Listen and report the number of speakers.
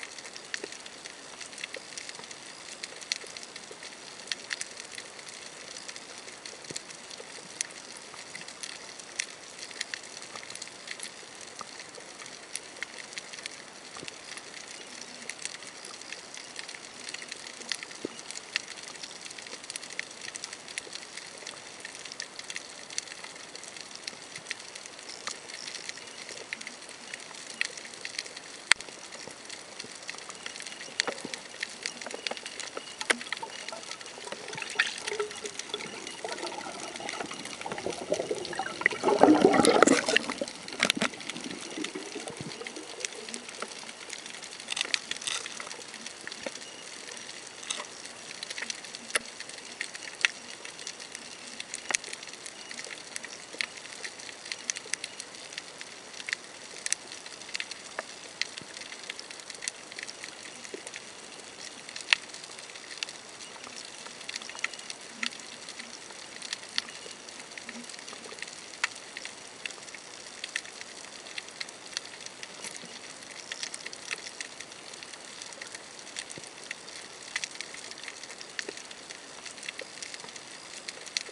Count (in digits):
0